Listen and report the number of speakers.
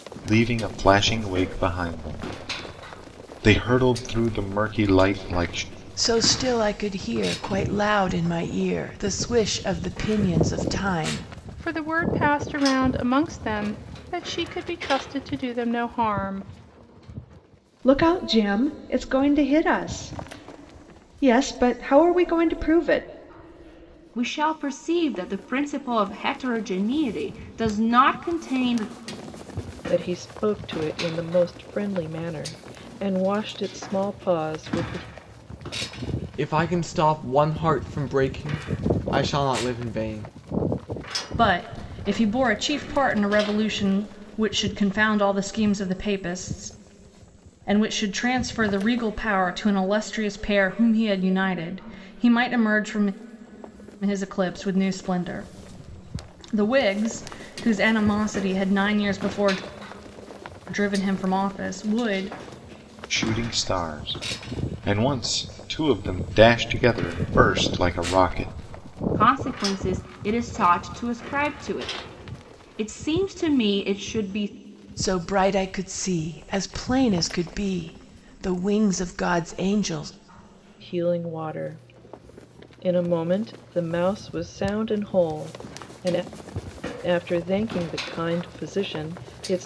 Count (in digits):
8